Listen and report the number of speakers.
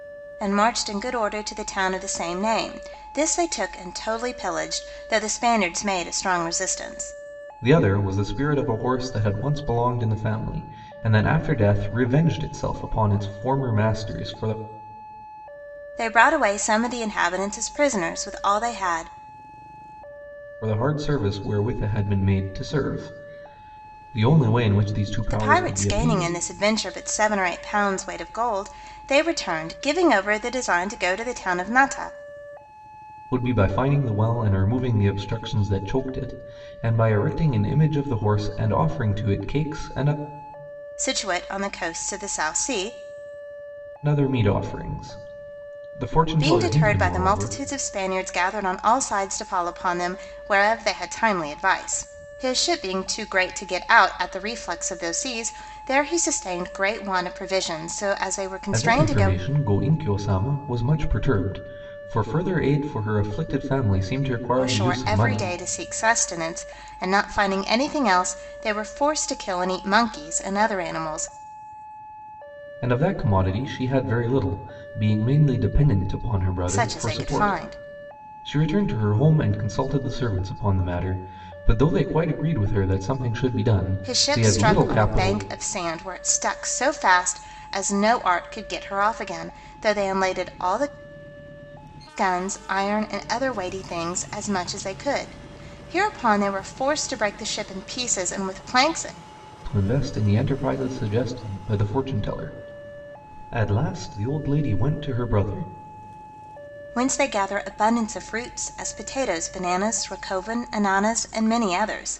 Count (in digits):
2